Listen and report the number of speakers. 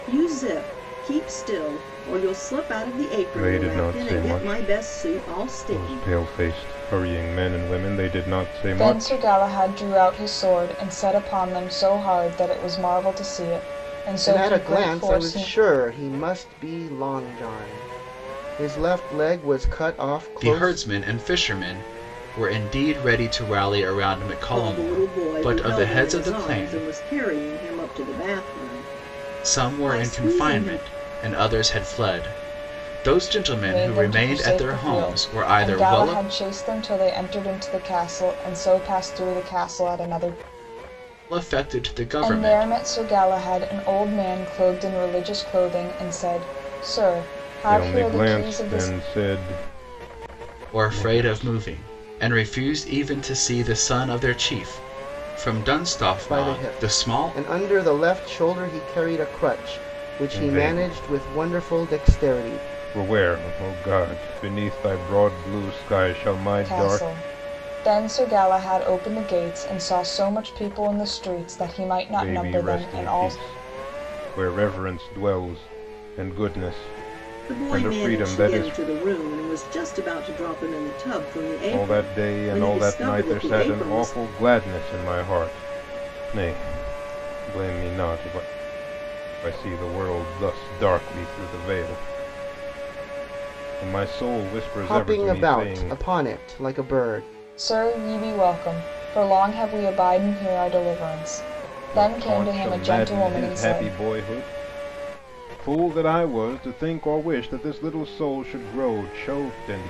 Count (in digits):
5